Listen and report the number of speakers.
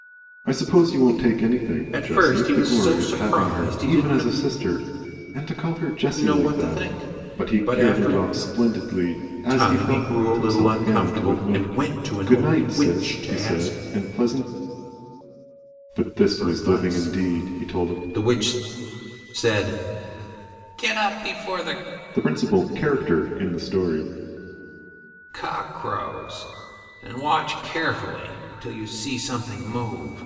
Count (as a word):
two